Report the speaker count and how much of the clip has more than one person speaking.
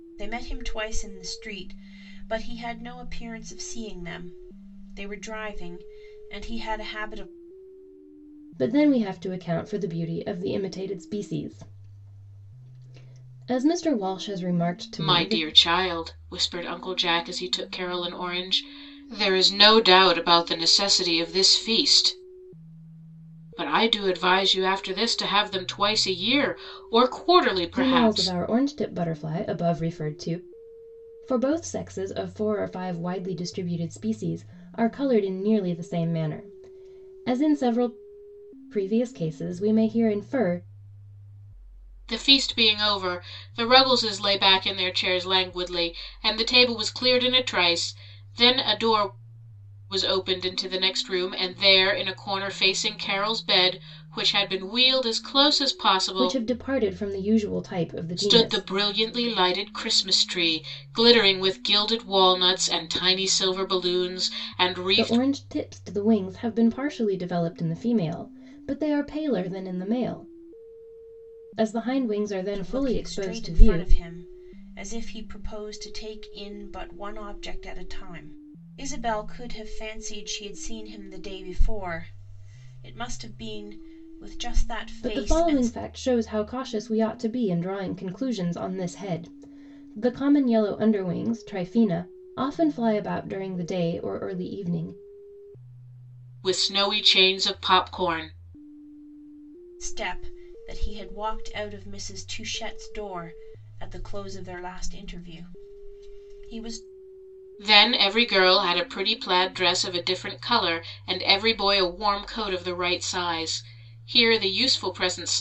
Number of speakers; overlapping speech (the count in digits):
3, about 4%